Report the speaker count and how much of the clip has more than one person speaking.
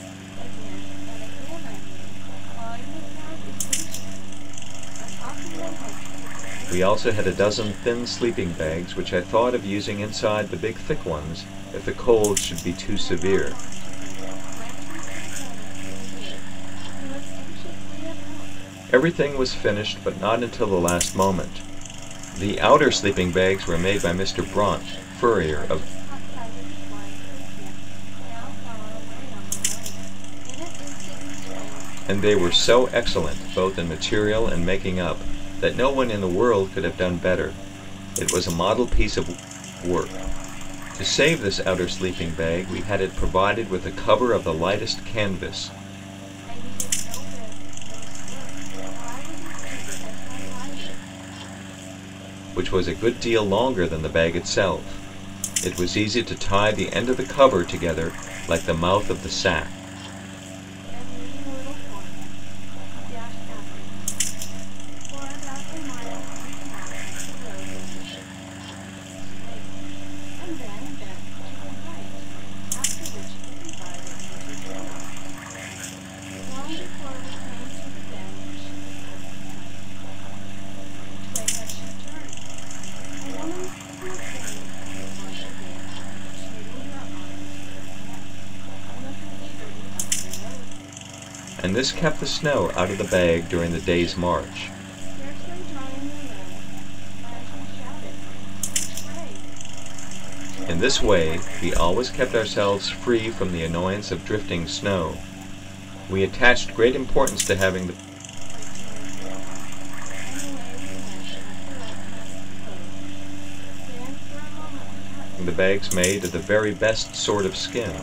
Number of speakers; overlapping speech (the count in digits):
2, about 4%